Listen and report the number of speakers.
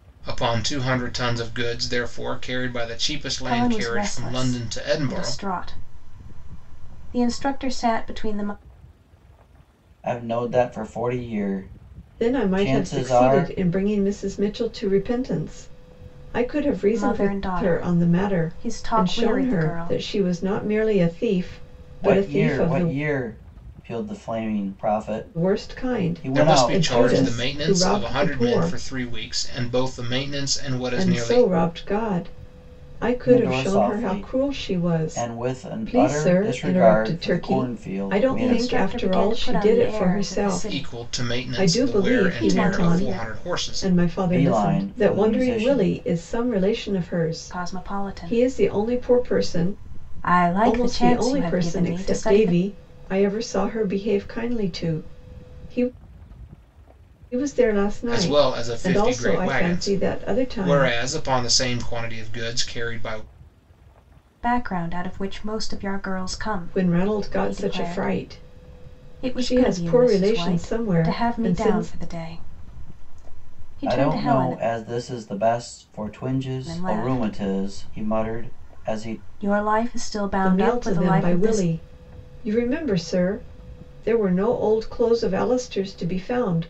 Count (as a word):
four